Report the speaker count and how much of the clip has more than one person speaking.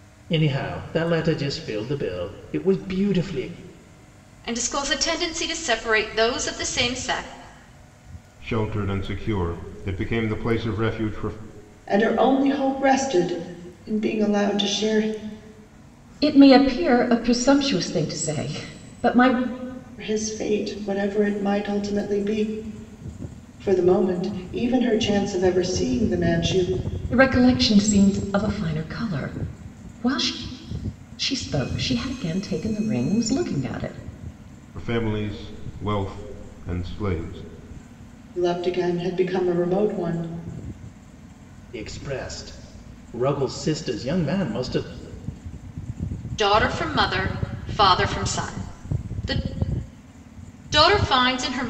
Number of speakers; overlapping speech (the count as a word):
five, no overlap